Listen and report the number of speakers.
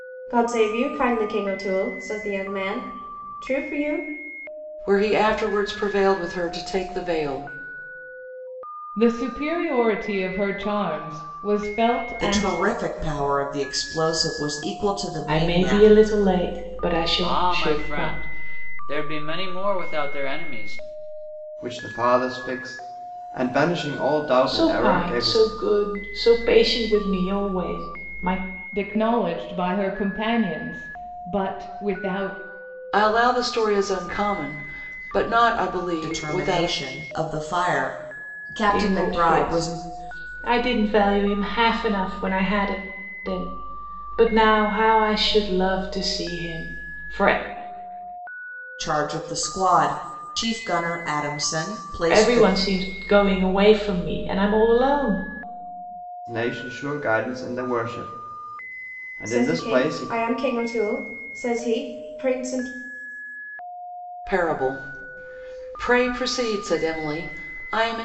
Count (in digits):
7